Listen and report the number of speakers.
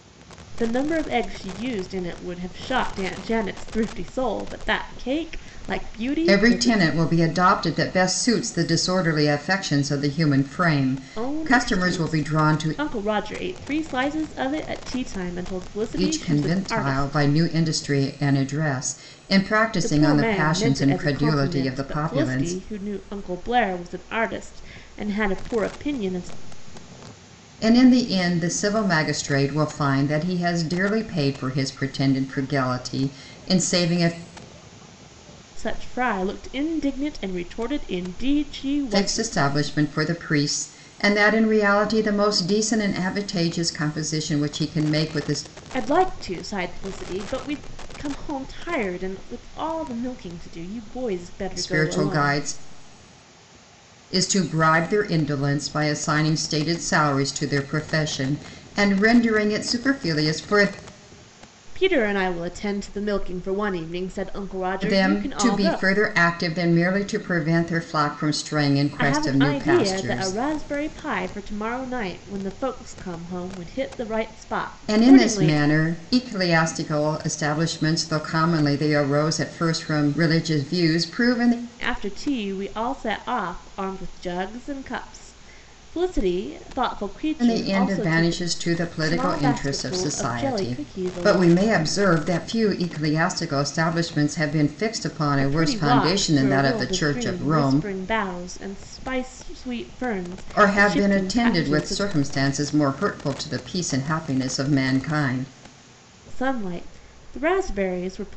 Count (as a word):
two